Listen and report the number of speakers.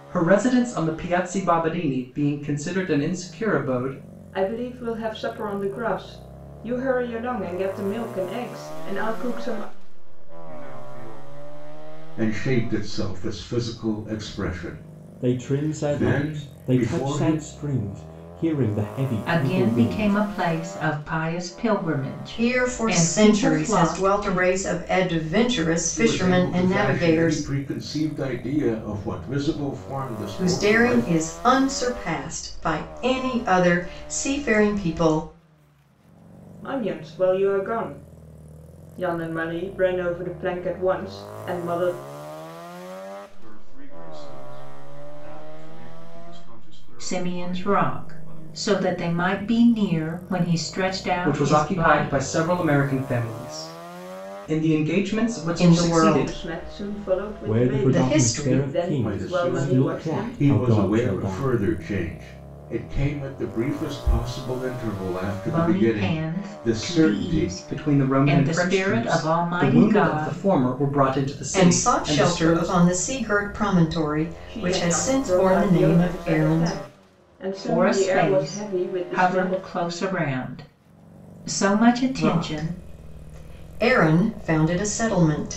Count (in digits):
7